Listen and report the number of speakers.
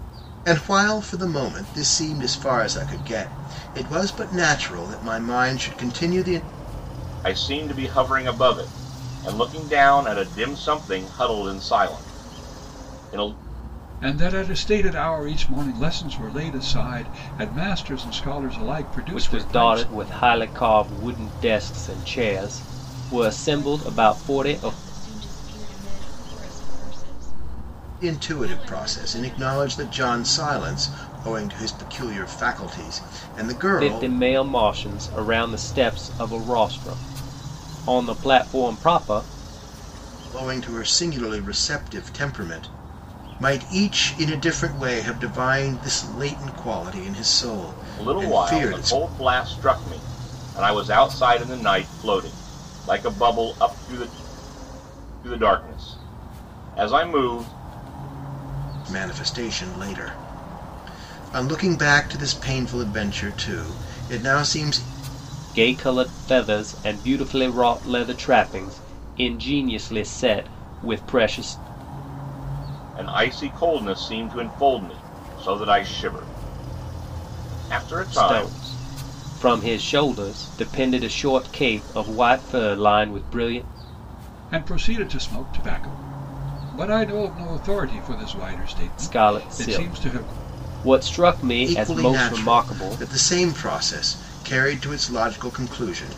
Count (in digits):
5